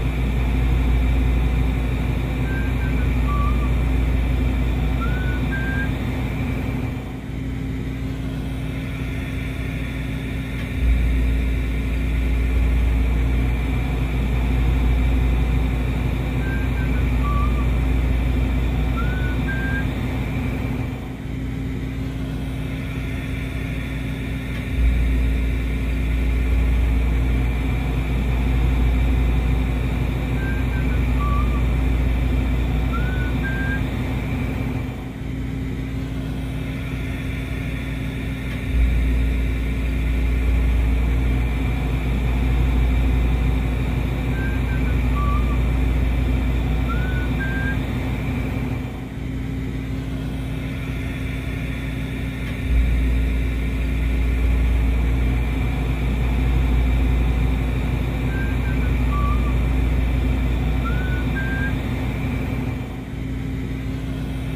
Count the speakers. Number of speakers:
0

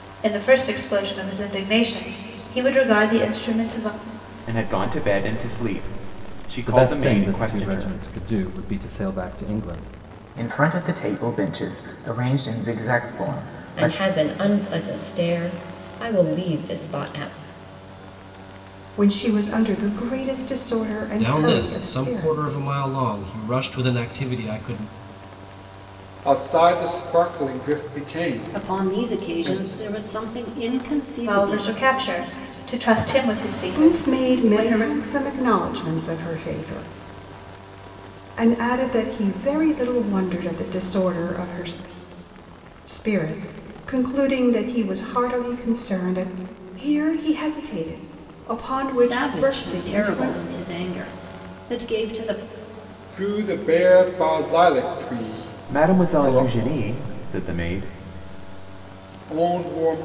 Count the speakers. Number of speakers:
9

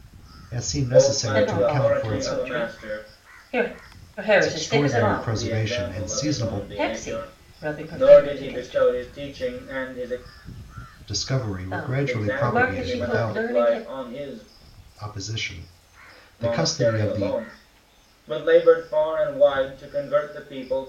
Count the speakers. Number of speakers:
3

